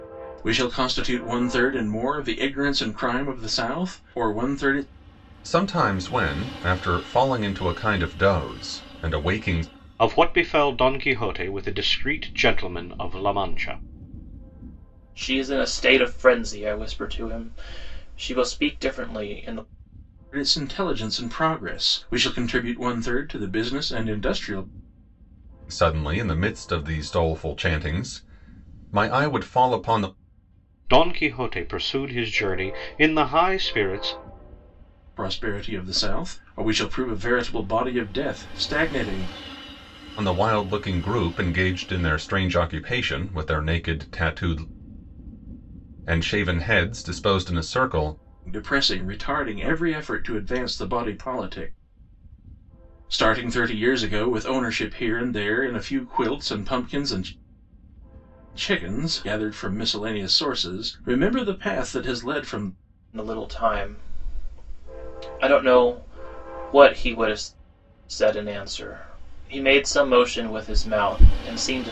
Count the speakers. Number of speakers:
4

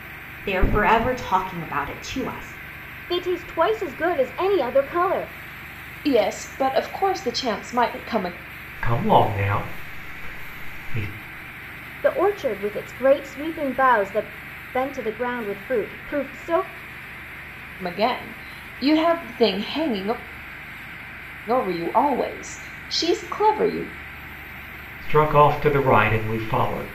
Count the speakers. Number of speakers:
4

